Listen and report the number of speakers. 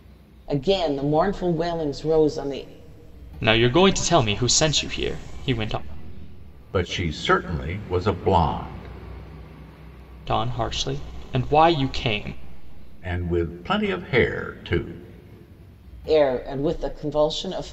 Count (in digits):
3